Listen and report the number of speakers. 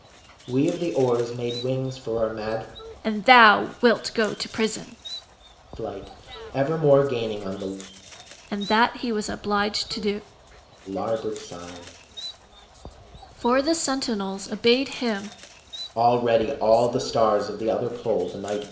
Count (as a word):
two